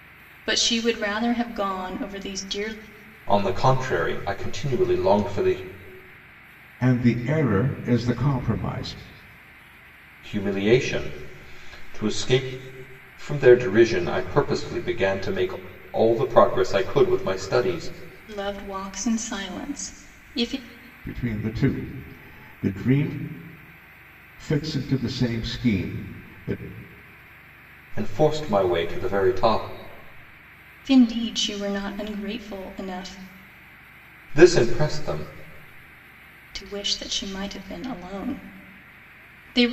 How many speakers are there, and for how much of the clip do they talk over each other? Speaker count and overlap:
three, no overlap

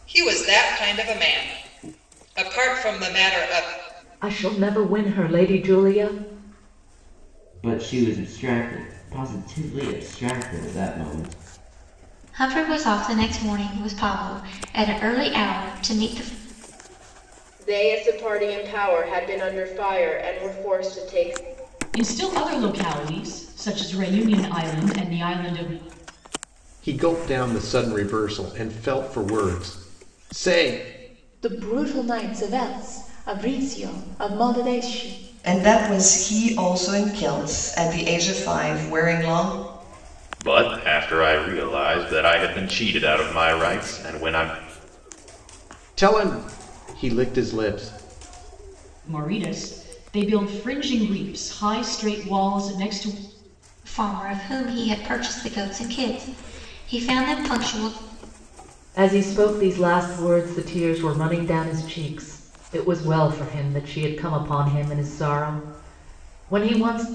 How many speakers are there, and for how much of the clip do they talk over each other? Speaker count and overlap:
ten, no overlap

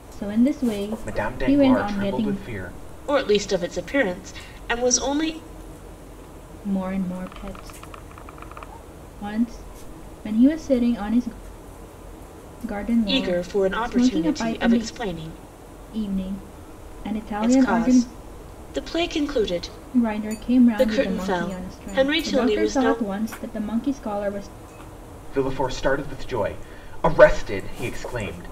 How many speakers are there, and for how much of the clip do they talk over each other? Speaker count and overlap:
three, about 22%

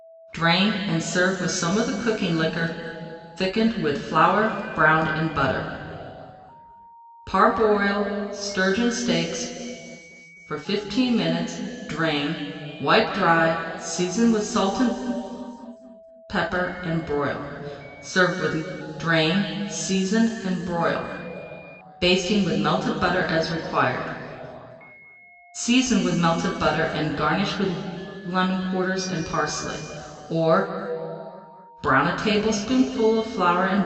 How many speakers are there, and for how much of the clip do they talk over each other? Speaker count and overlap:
one, no overlap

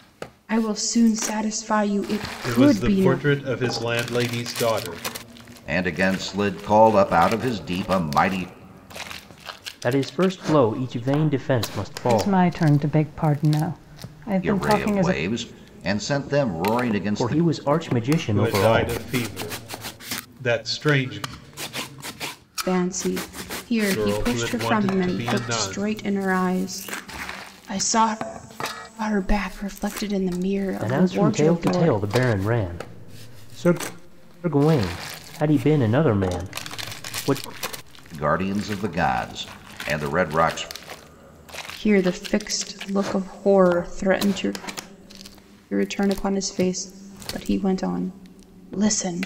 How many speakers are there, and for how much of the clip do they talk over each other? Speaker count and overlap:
five, about 13%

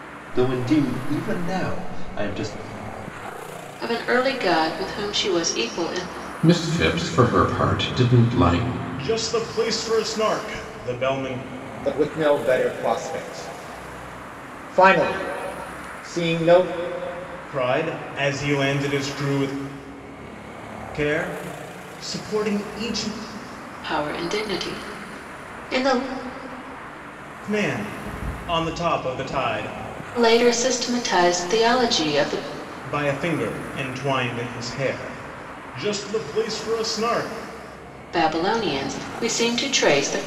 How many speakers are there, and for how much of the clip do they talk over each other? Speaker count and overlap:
five, no overlap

